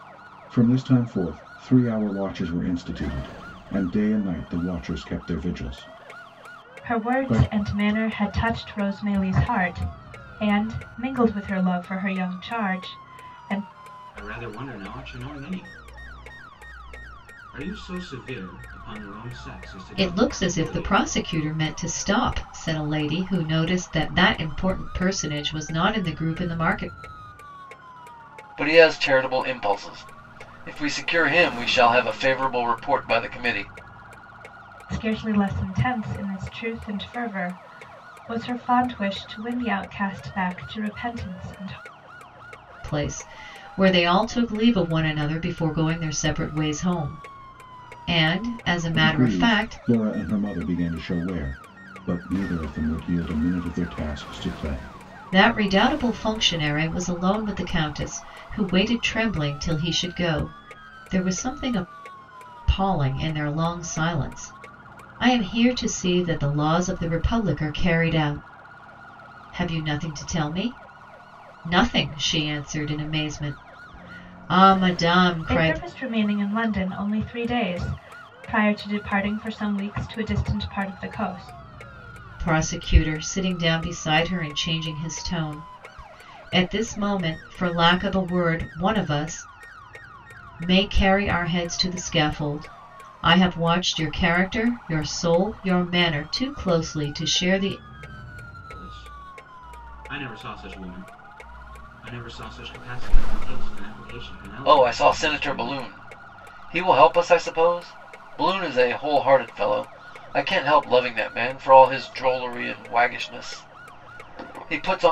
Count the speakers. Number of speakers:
five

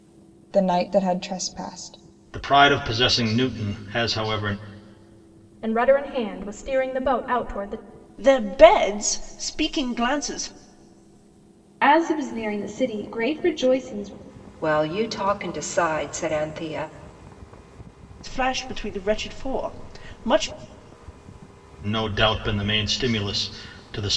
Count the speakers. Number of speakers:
six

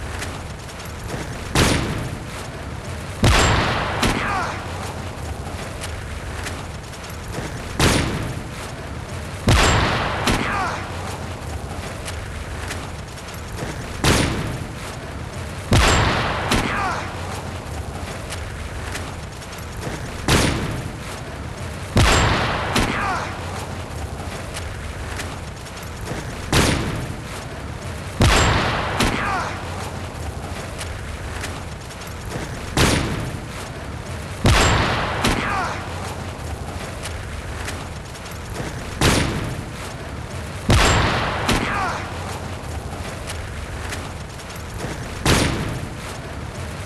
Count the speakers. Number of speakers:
zero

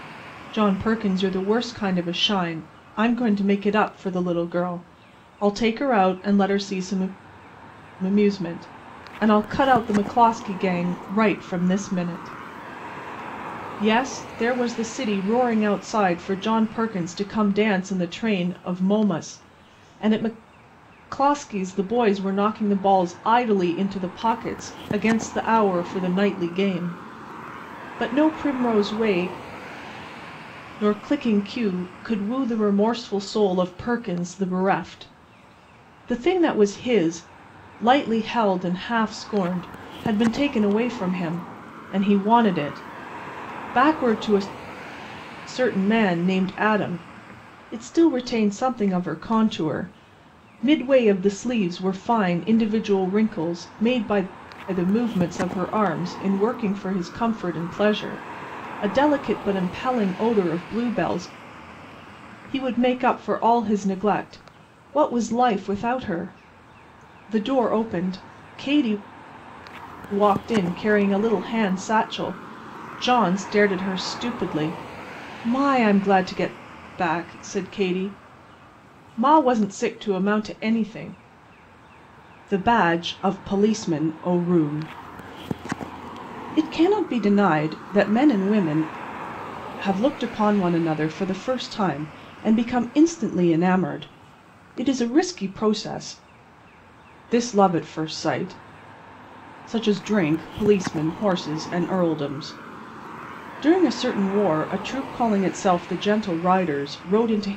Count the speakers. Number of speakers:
one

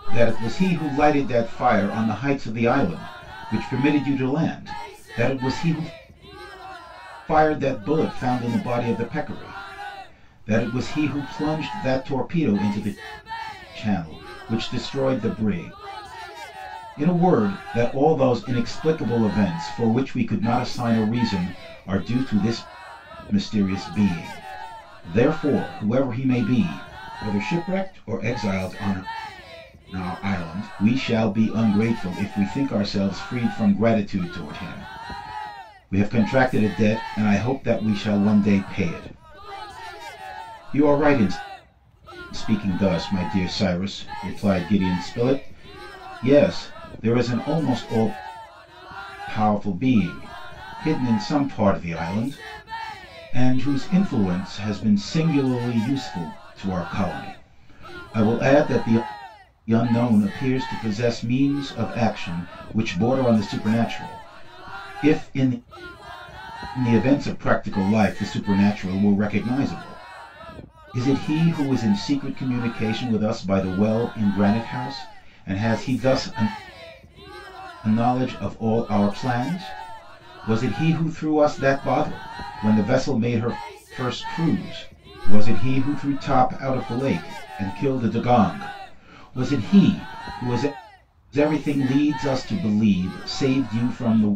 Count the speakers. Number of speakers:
one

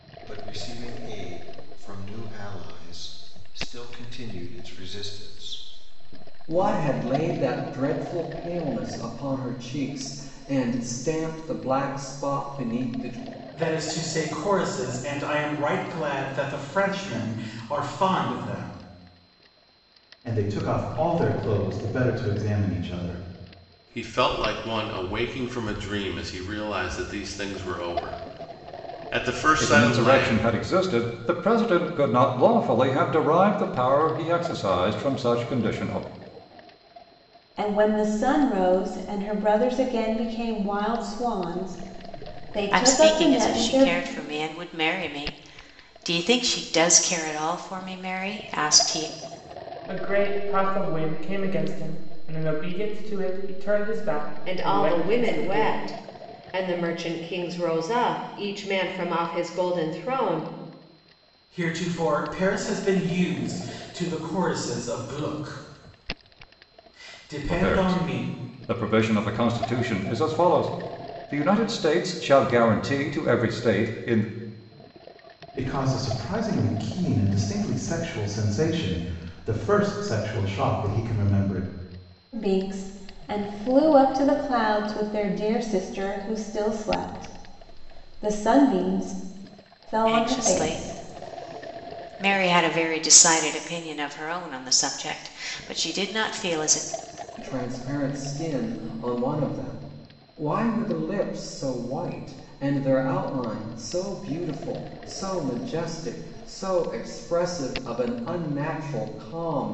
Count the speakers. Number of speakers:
ten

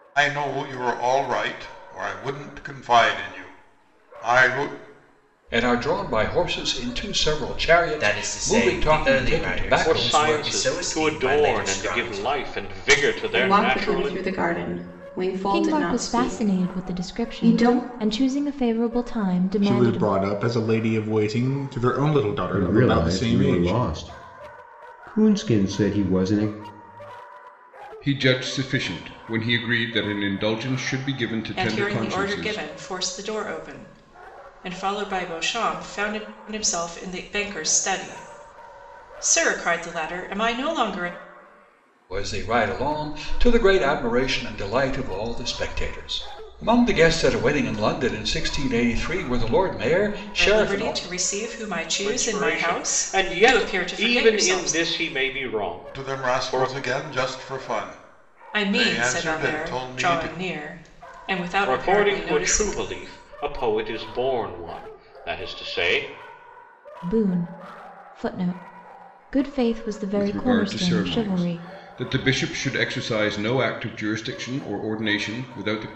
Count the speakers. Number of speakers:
ten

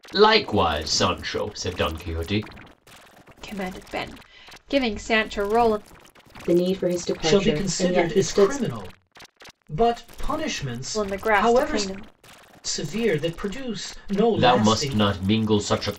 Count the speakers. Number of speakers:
four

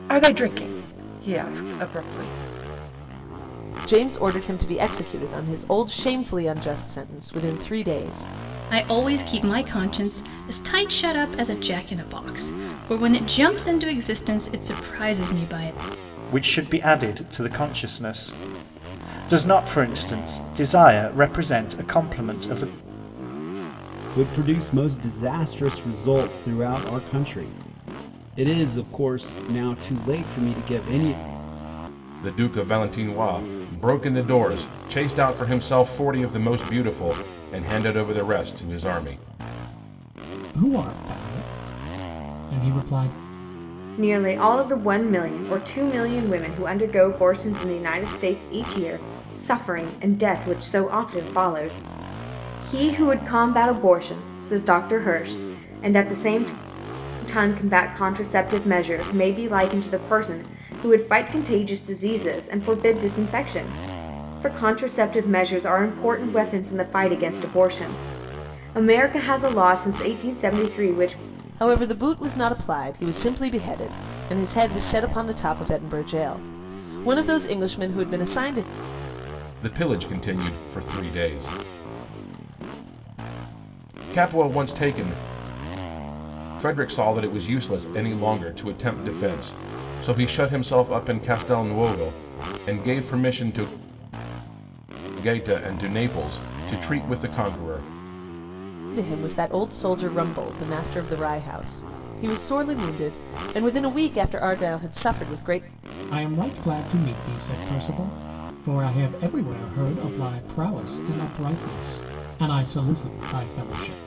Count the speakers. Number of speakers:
eight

